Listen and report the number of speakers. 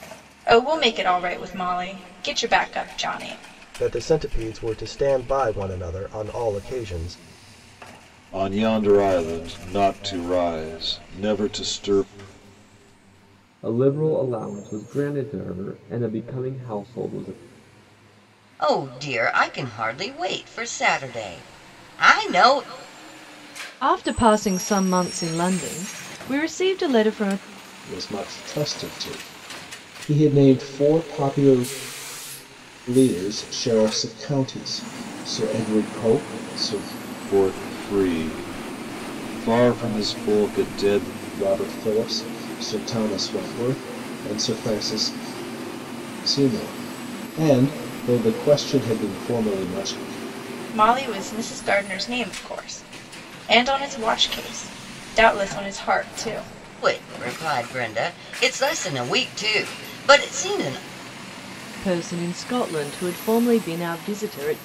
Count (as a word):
seven